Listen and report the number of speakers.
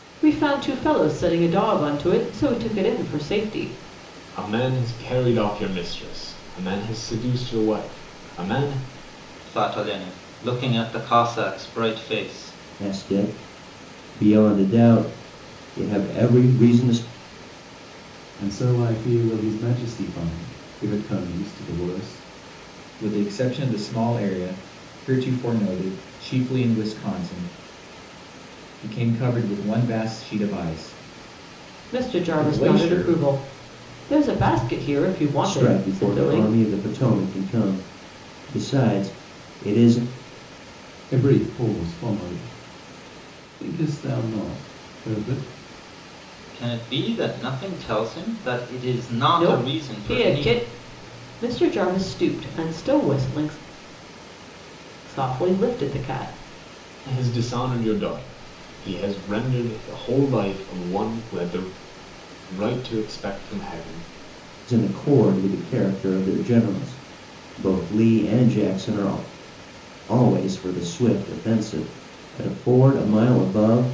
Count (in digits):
6